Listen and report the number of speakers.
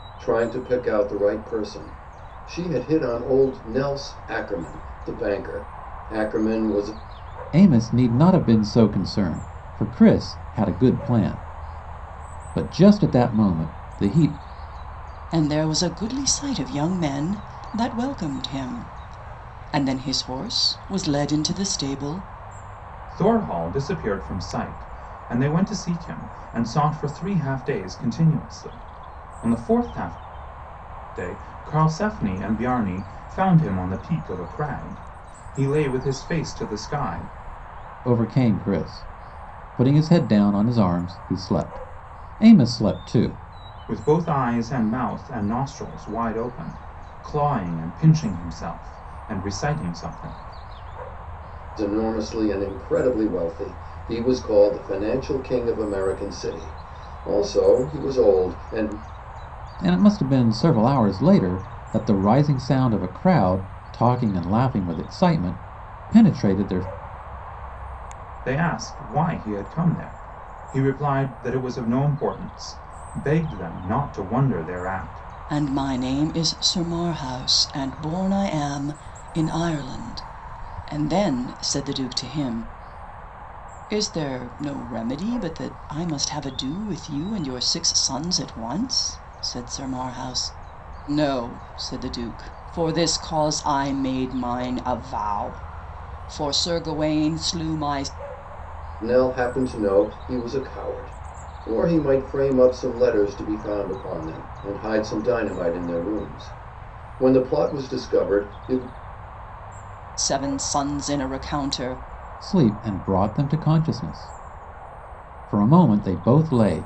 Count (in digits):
4